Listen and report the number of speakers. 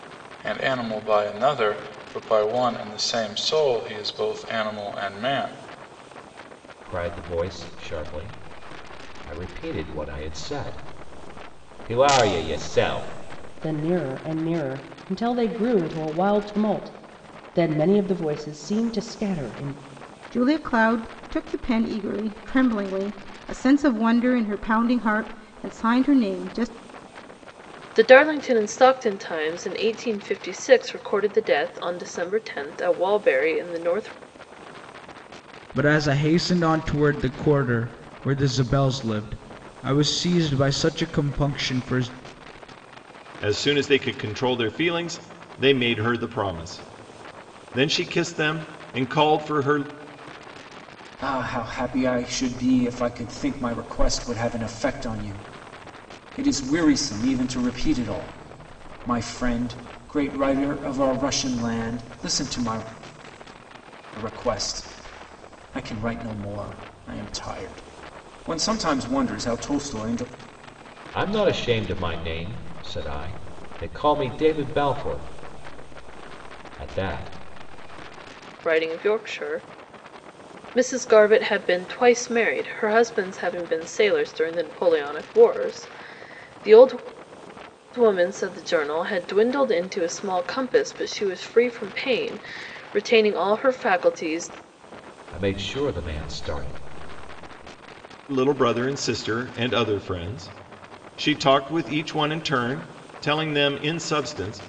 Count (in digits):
8